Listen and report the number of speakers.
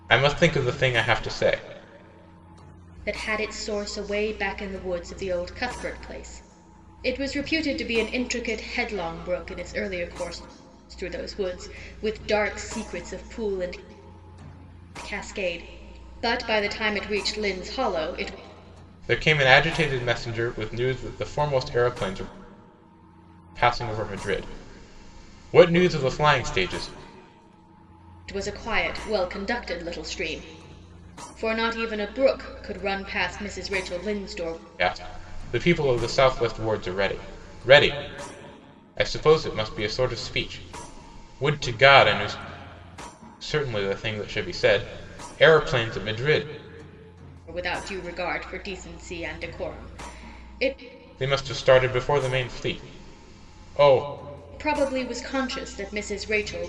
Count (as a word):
two